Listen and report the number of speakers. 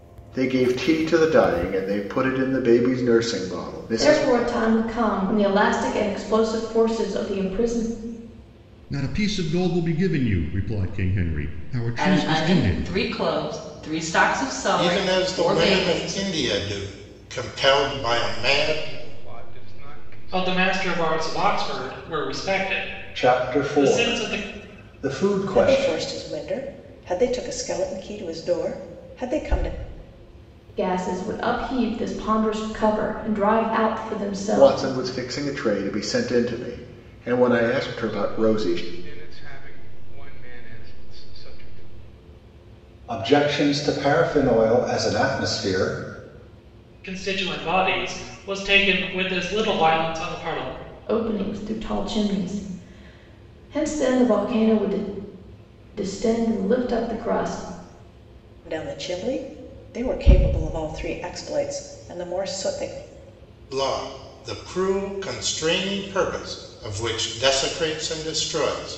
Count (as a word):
nine